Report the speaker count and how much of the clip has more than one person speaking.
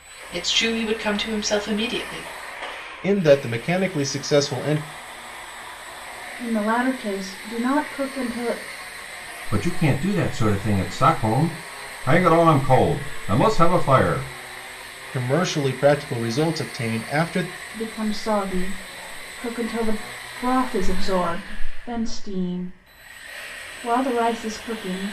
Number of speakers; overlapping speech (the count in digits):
4, no overlap